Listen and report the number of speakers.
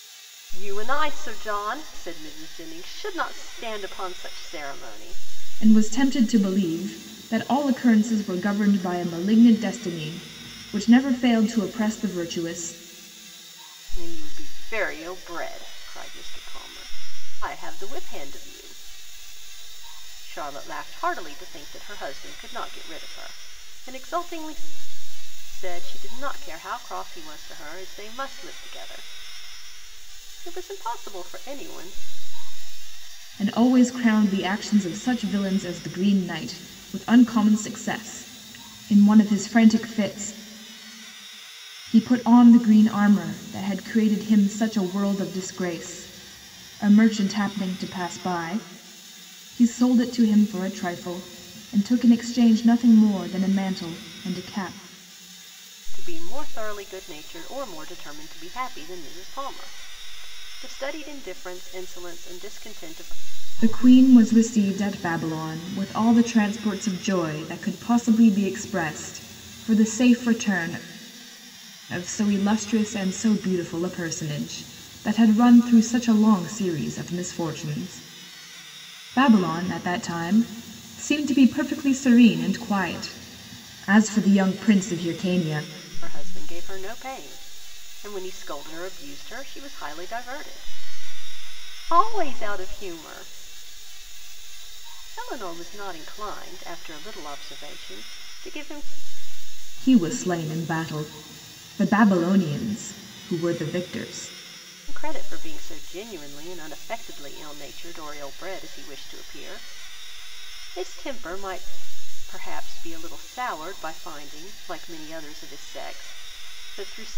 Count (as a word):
two